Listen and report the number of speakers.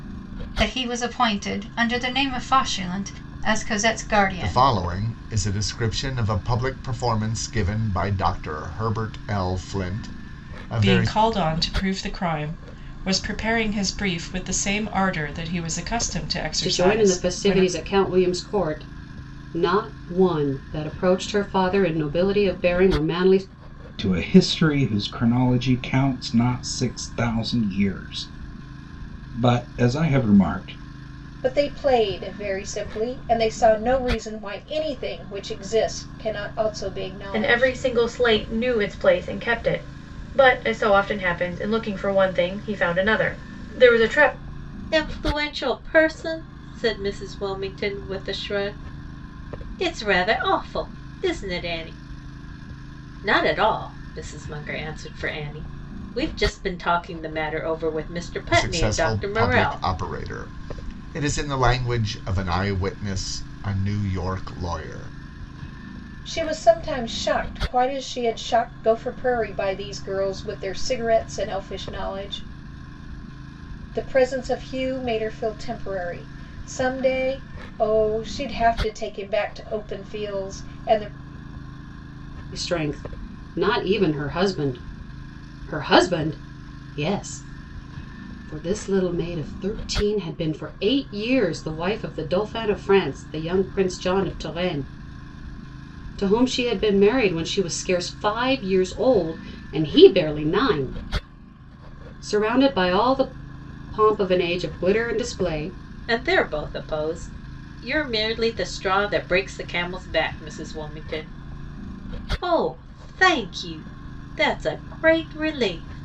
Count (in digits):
8